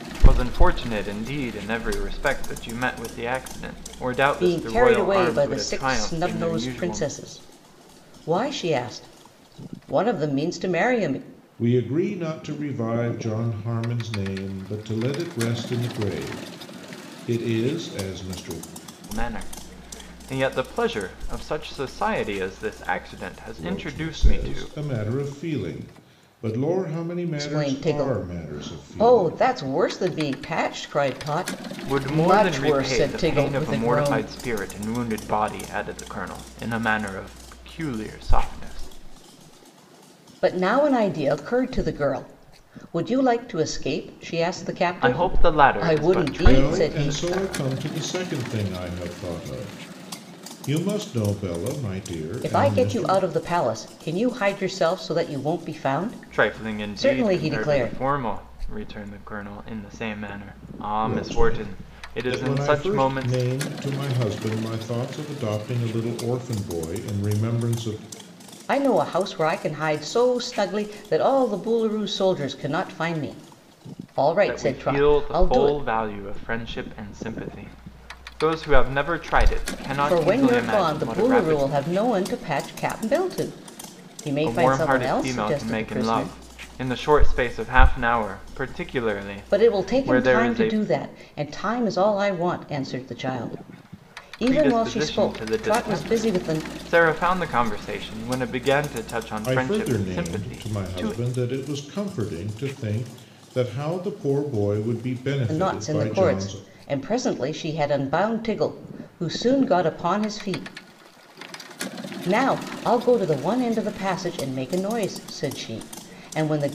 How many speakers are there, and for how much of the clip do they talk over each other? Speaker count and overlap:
3, about 24%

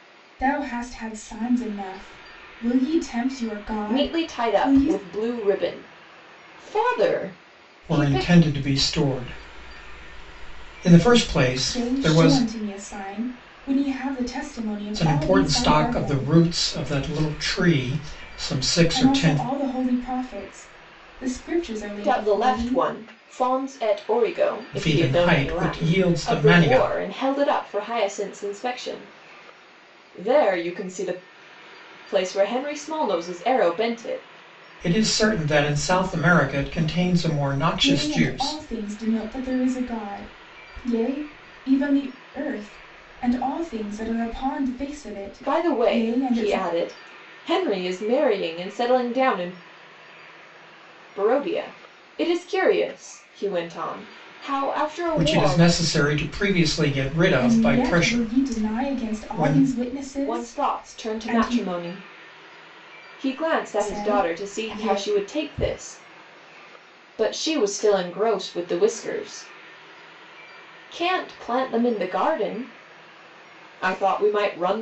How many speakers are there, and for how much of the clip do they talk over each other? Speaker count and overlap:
3, about 20%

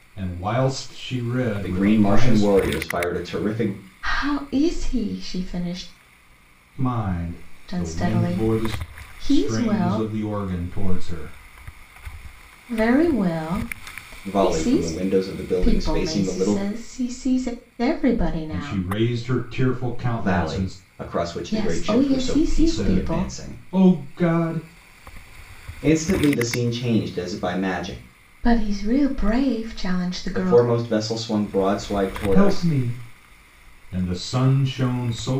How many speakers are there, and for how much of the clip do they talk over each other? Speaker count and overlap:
3, about 24%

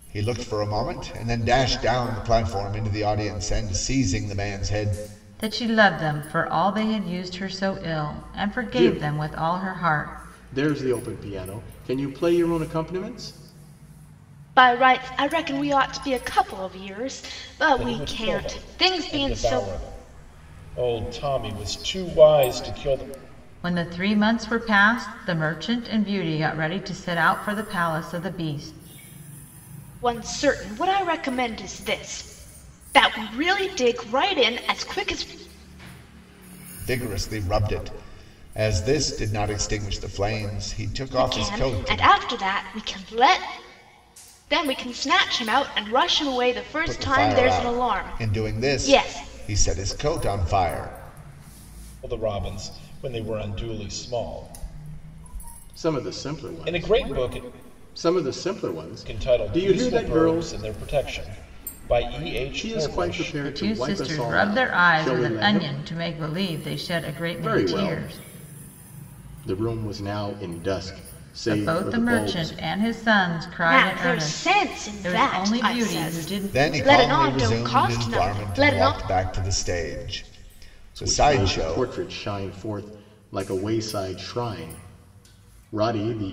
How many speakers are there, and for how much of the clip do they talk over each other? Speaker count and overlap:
5, about 25%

